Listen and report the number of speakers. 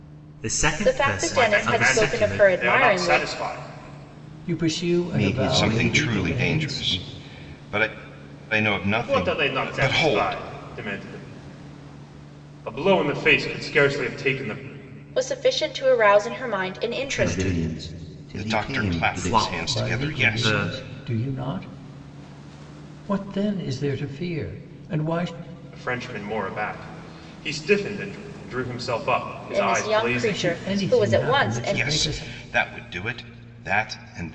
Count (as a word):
six